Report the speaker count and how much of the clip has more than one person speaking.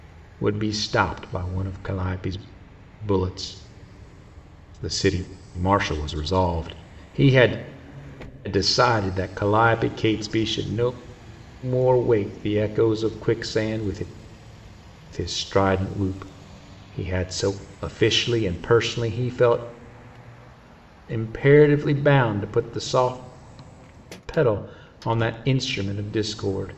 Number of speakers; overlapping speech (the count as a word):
one, no overlap